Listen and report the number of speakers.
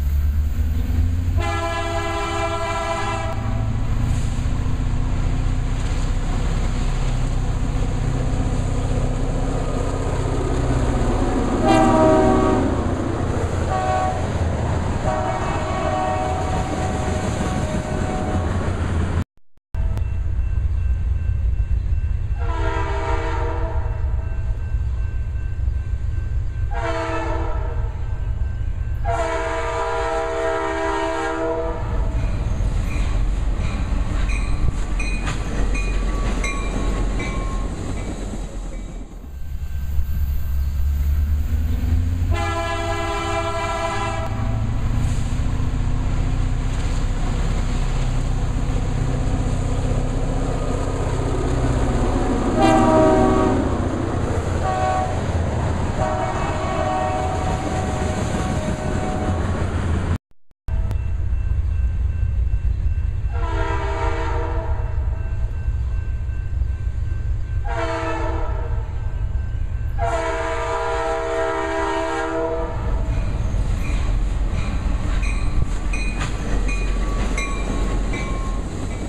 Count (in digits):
0